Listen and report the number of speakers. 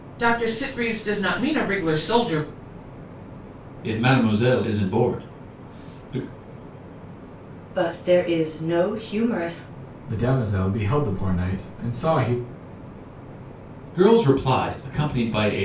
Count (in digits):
4